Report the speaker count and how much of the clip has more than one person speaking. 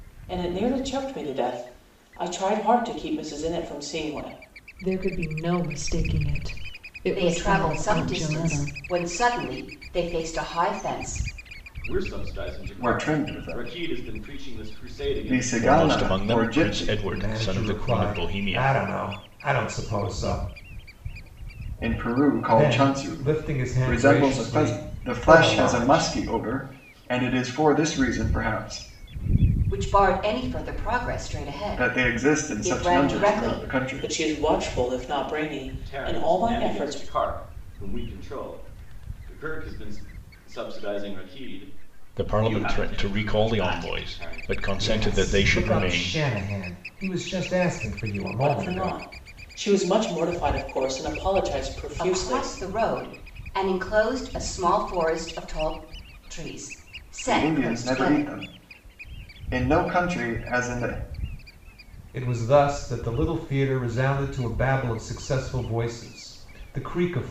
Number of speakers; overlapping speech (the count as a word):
seven, about 31%